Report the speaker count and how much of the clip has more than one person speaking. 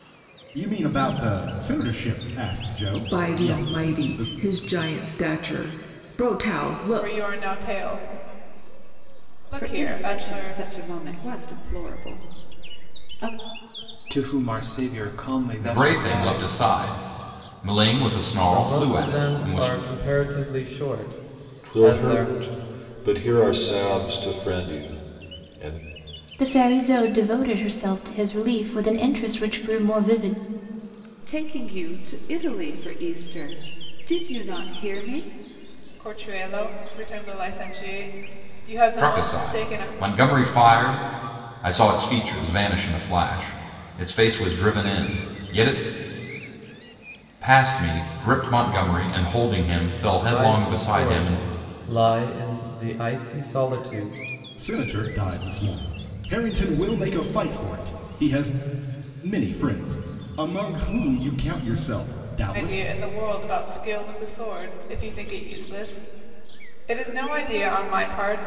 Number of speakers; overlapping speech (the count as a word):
nine, about 12%